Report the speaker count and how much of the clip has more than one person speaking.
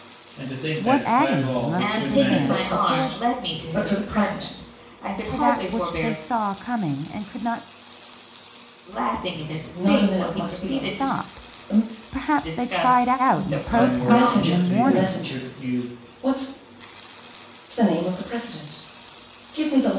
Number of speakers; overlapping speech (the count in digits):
4, about 51%